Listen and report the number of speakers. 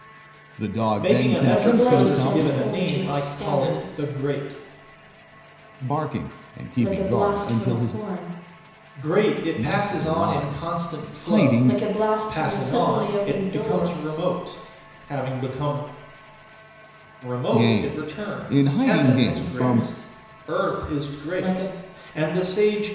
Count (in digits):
3